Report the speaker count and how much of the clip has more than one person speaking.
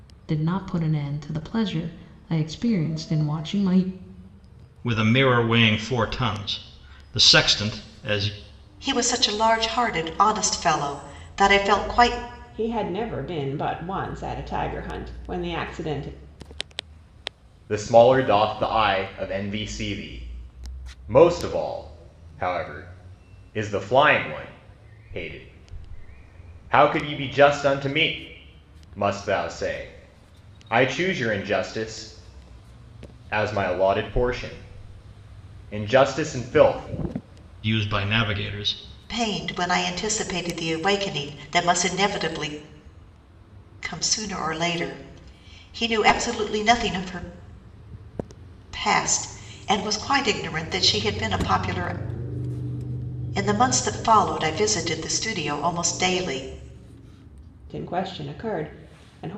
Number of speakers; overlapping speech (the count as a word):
five, no overlap